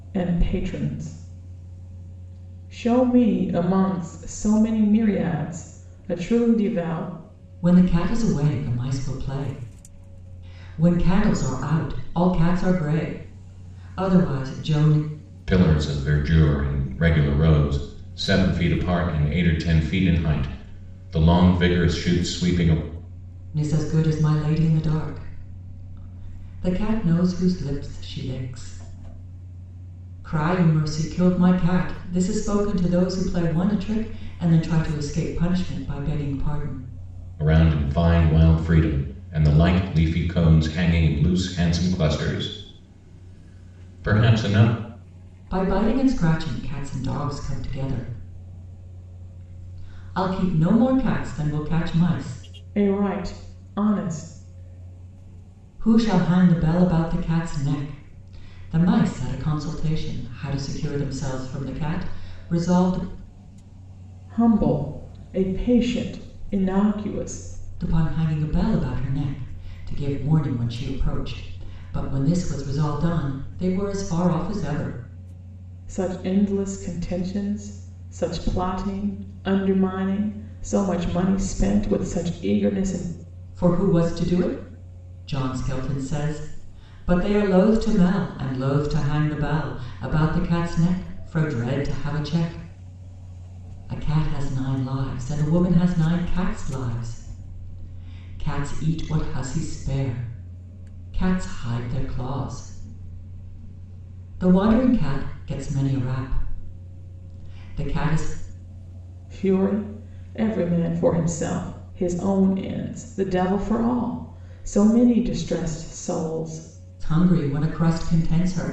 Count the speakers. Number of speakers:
three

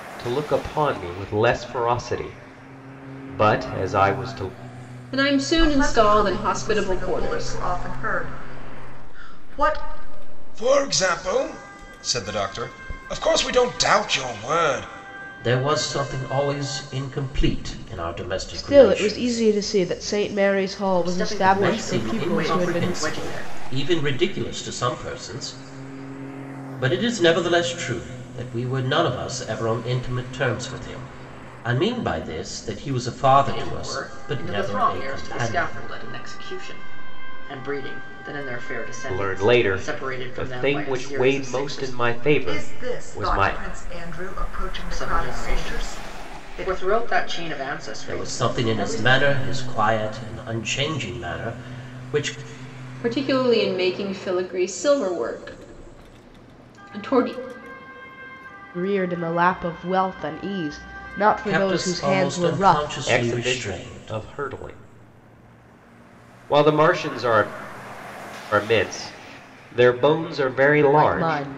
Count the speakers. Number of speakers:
seven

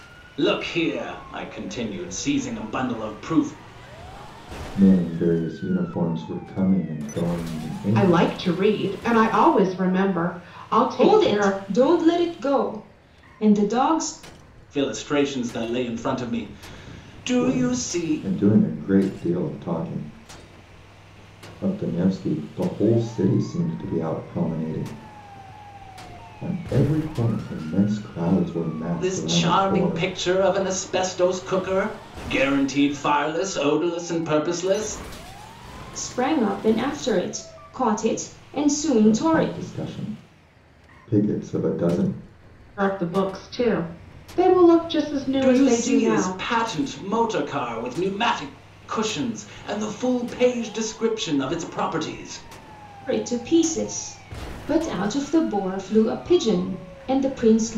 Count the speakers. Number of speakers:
four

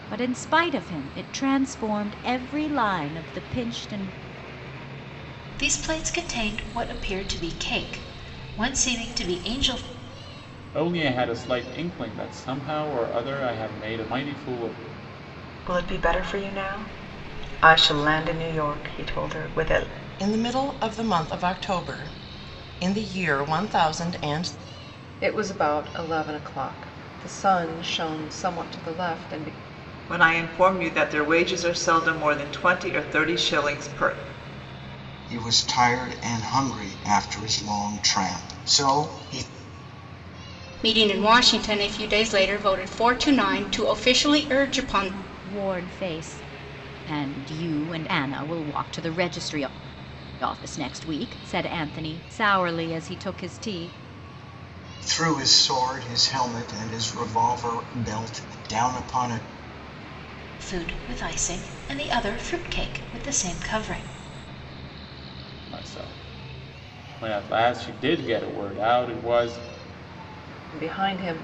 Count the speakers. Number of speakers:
nine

